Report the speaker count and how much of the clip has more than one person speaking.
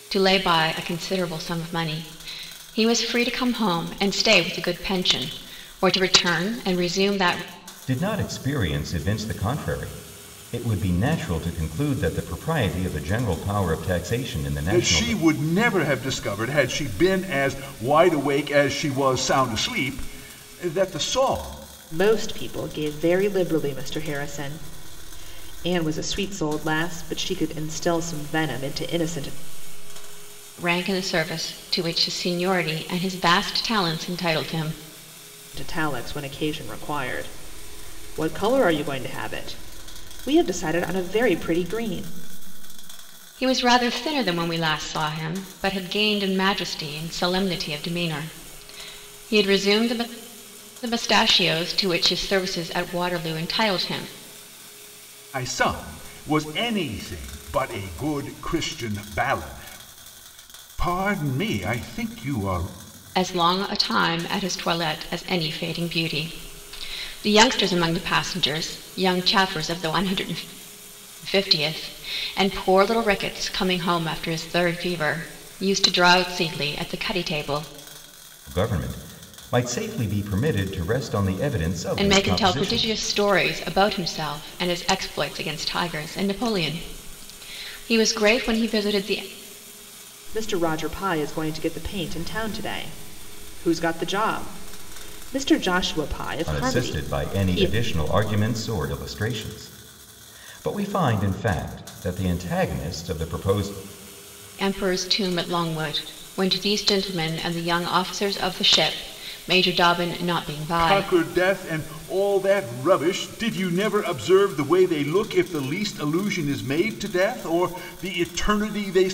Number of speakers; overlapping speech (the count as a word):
four, about 3%